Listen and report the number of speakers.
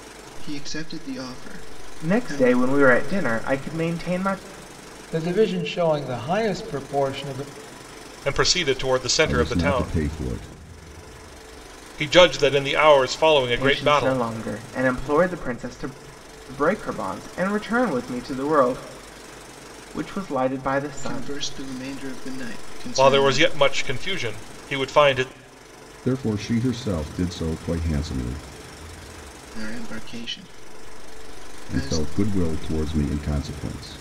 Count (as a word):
five